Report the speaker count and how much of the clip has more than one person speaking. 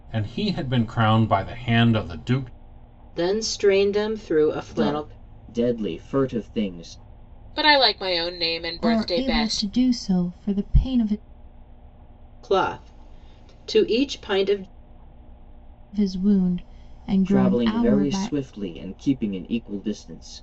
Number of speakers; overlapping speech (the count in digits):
5, about 13%